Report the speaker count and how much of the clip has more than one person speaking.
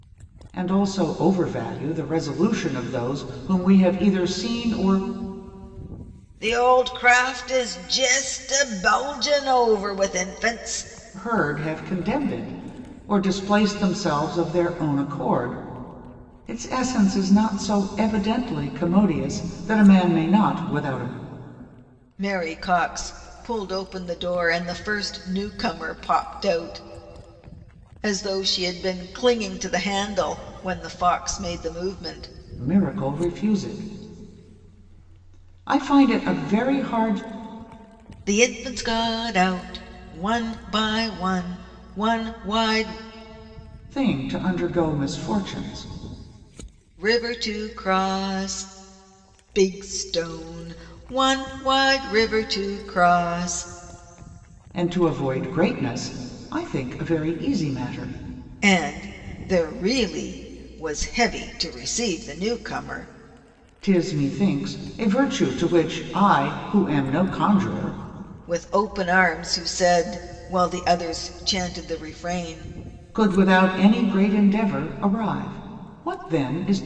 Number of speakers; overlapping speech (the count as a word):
two, no overlap